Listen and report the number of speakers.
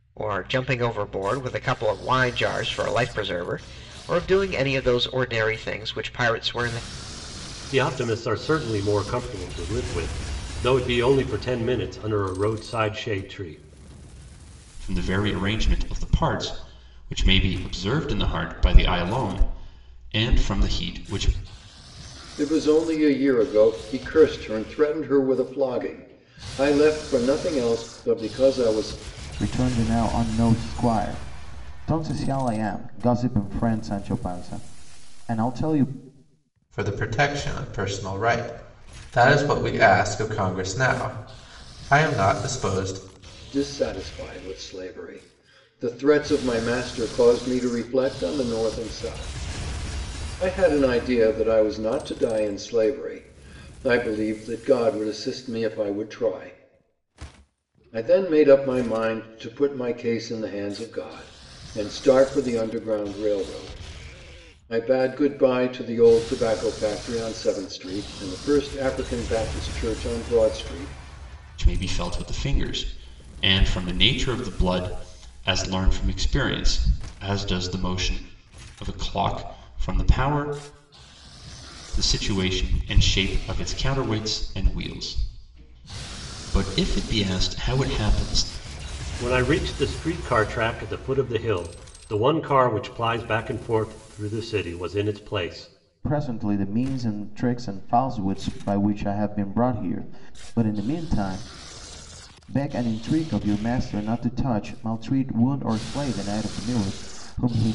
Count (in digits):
6